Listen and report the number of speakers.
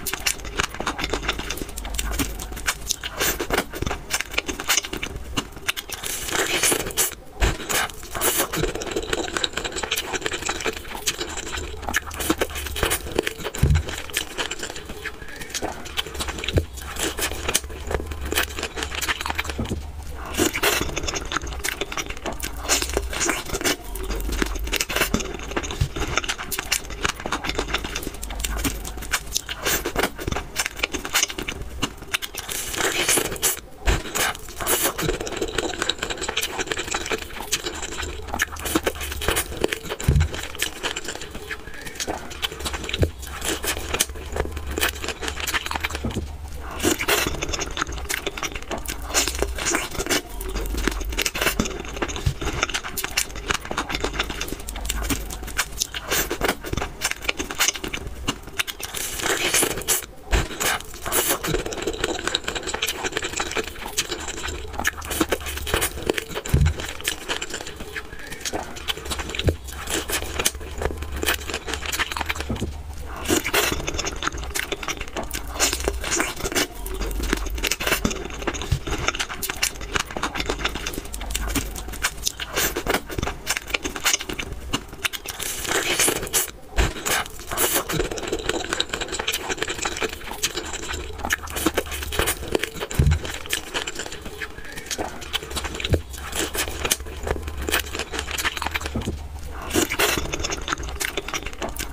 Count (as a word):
zero